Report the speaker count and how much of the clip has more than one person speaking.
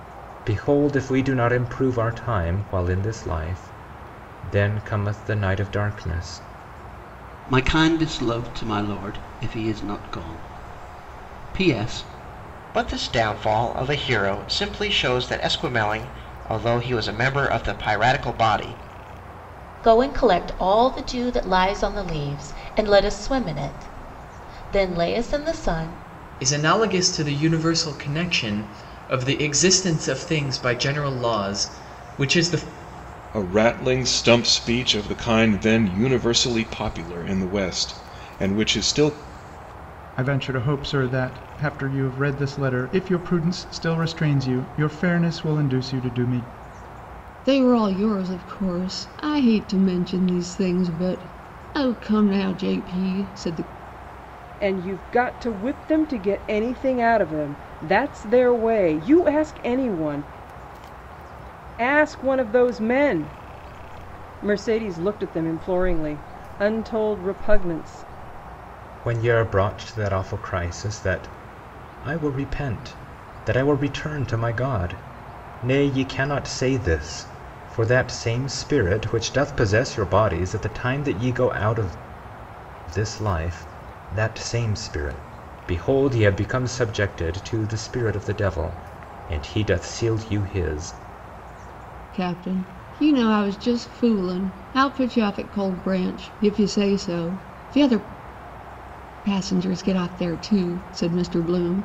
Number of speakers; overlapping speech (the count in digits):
9, no overlap